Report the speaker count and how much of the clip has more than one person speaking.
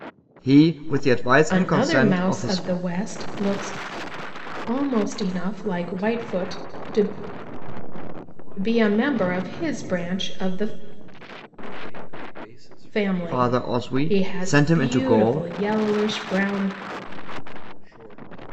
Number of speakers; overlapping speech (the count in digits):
3, about 52%